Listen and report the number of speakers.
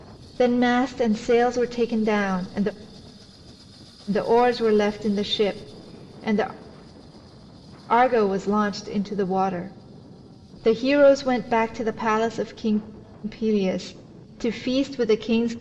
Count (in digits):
1